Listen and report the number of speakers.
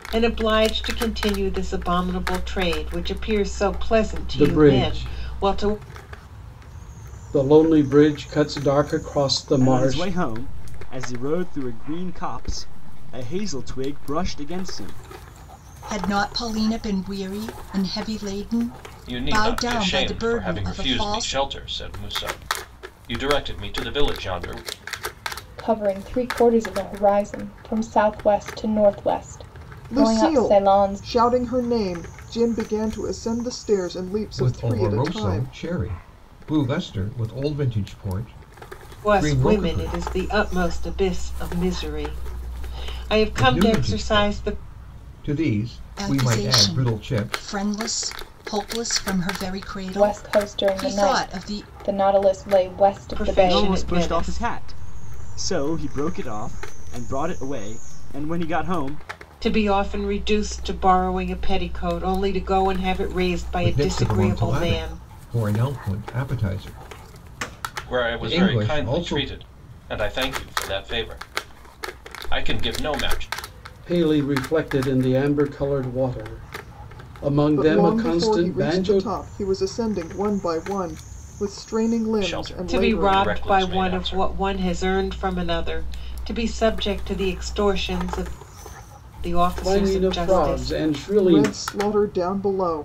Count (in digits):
8